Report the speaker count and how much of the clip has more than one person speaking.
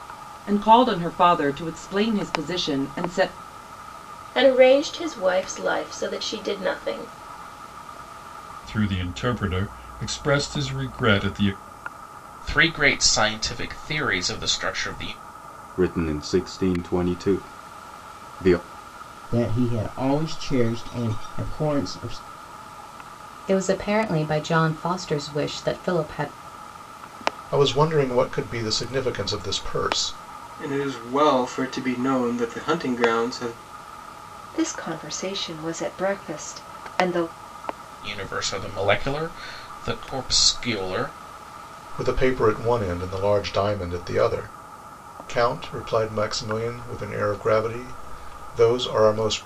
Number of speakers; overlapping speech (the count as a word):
ten, no overlap